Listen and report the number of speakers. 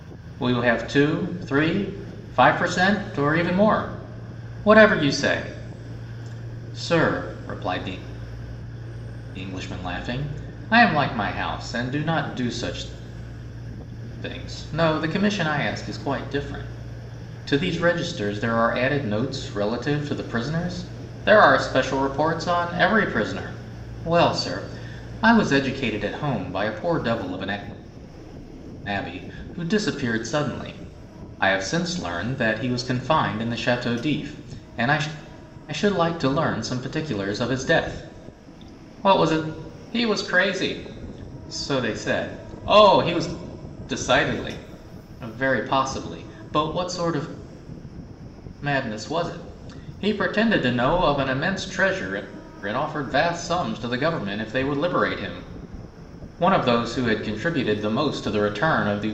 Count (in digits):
1